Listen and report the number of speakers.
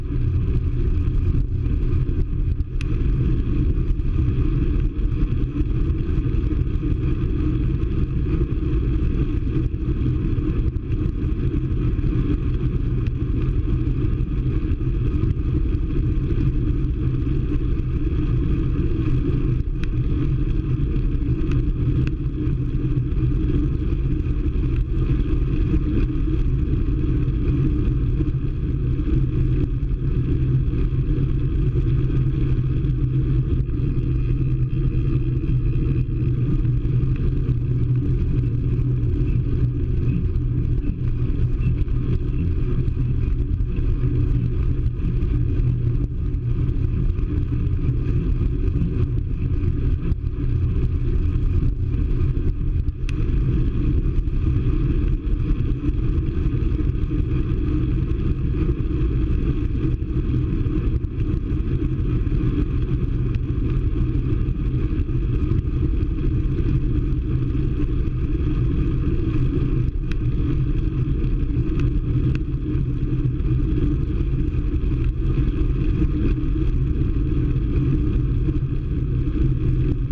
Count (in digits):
0